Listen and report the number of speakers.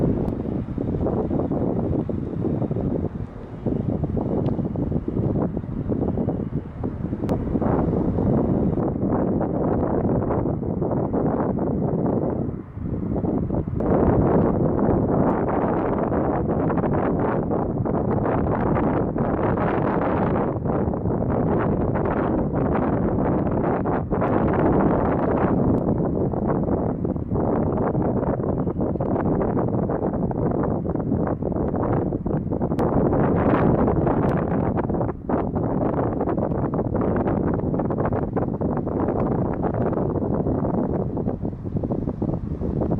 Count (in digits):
0